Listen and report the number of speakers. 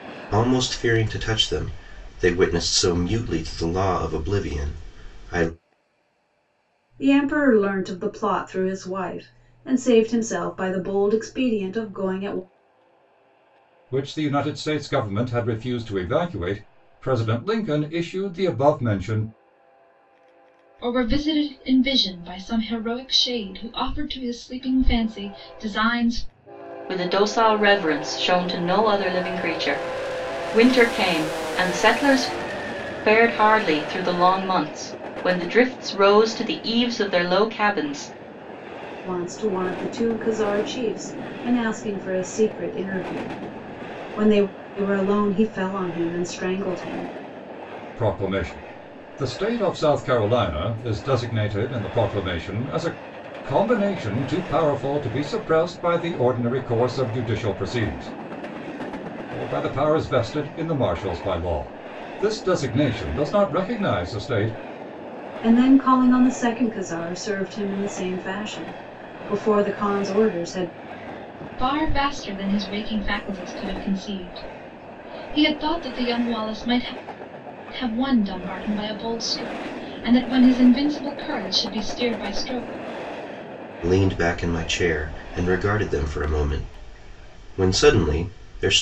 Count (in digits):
5